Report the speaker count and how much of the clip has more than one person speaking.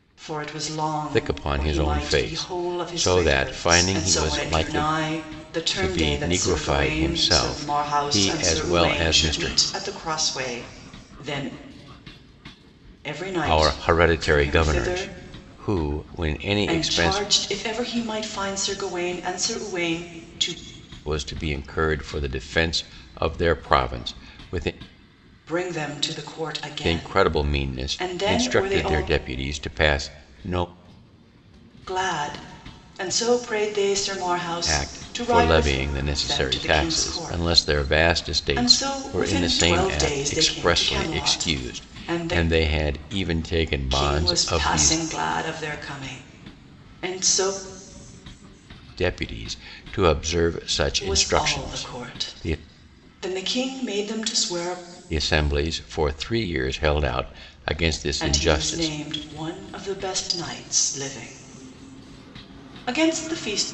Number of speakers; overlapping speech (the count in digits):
2, about 35%